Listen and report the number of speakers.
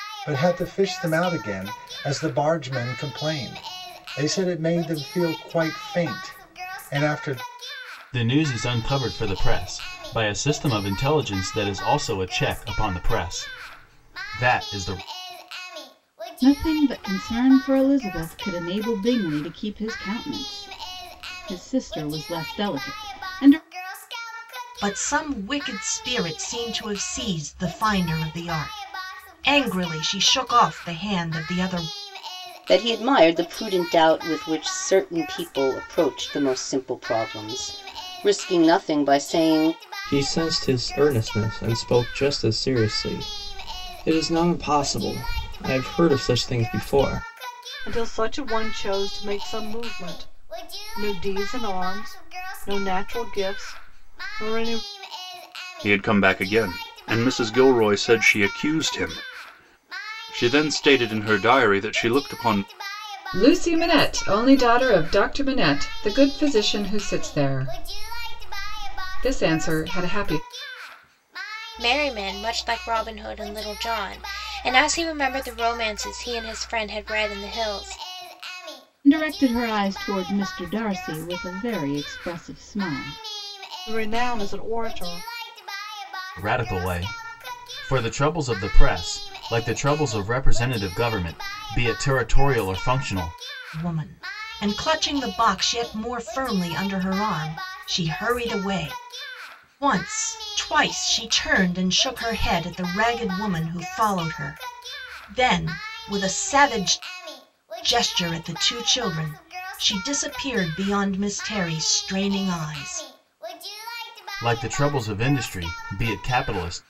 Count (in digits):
10